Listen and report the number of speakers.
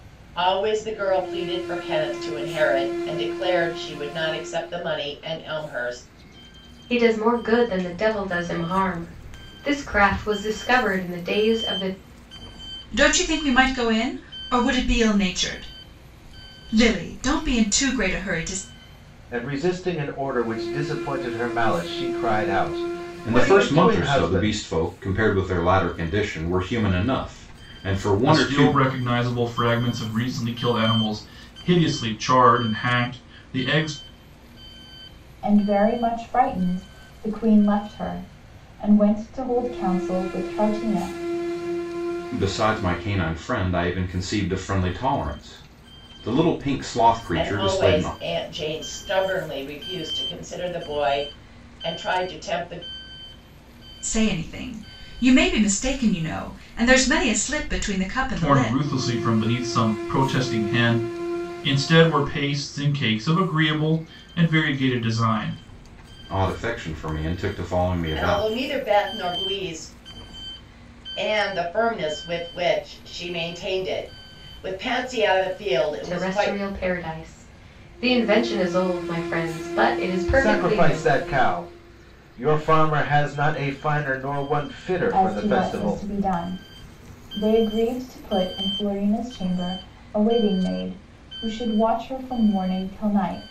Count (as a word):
seven